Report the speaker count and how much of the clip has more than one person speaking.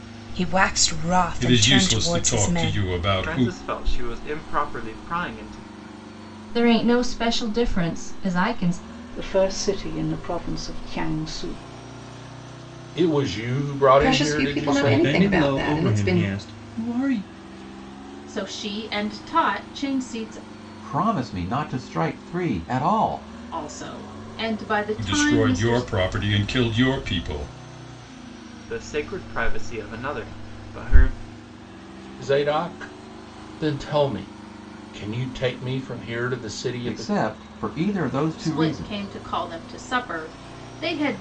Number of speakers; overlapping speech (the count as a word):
ten, about 15%